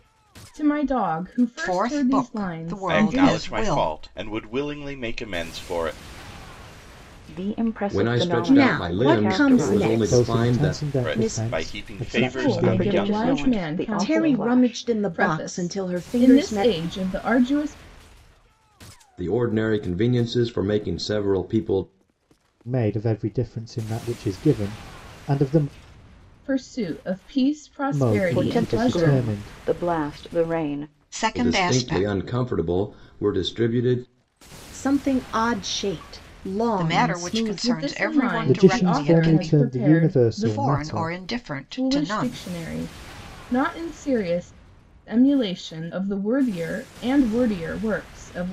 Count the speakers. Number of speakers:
7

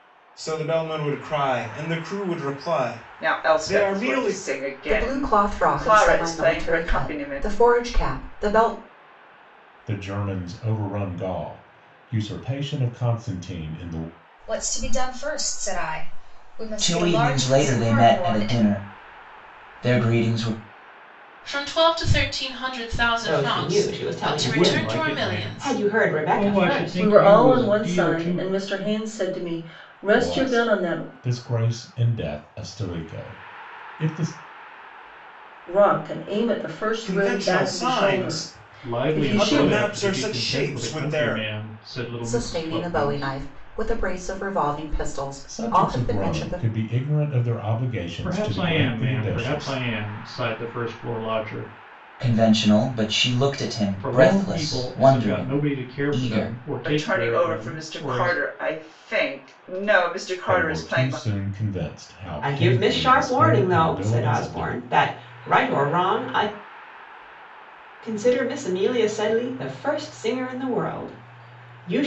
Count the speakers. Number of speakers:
10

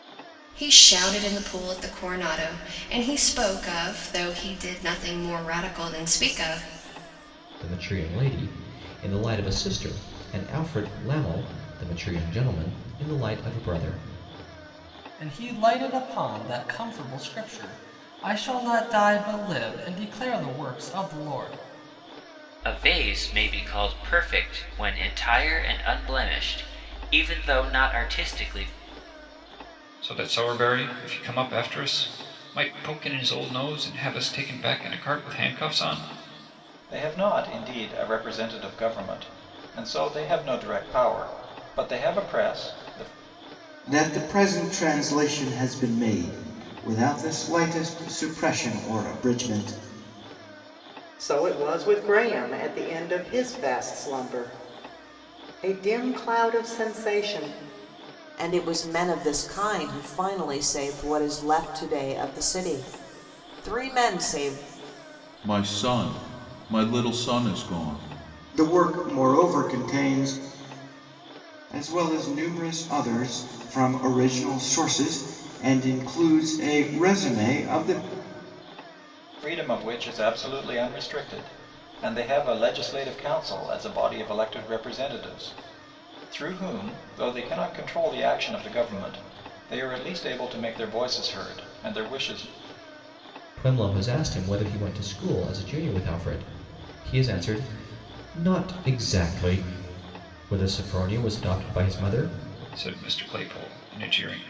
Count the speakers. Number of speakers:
10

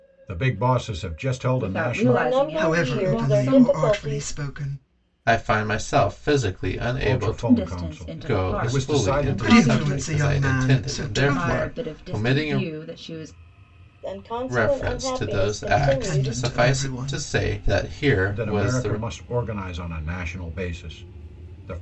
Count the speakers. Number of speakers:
5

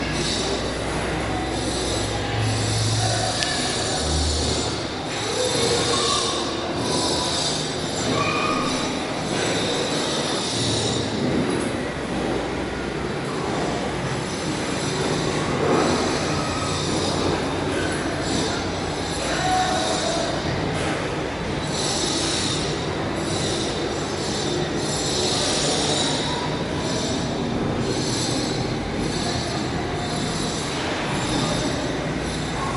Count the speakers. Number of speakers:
0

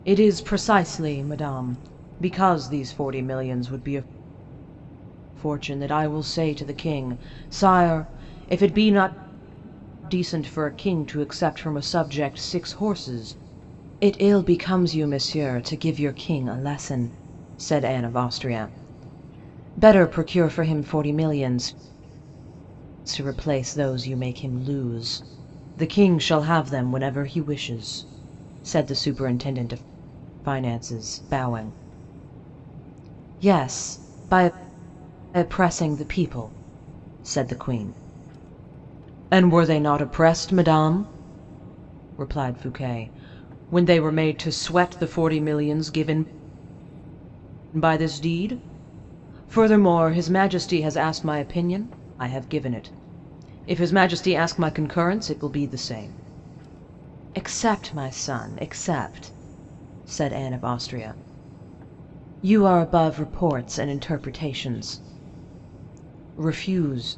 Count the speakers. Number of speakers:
1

